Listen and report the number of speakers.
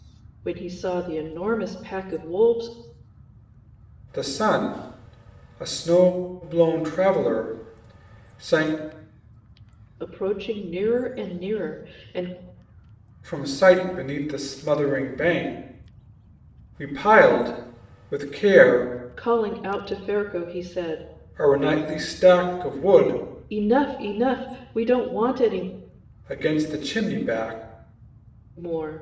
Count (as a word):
two